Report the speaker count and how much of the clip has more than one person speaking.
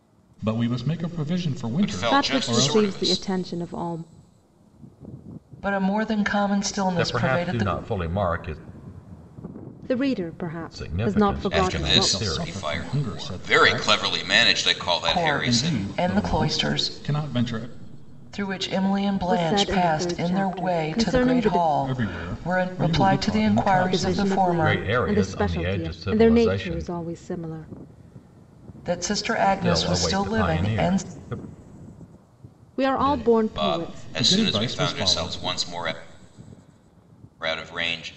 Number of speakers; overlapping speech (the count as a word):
five, about 50%